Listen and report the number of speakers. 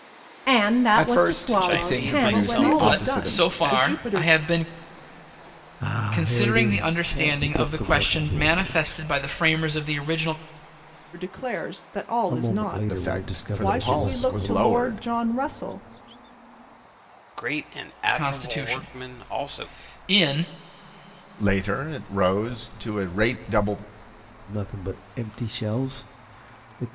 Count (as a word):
six